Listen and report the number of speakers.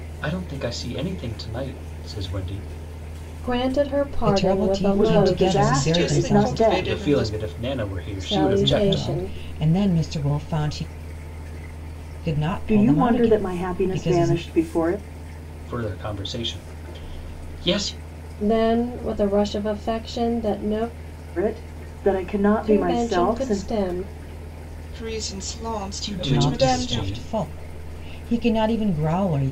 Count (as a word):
five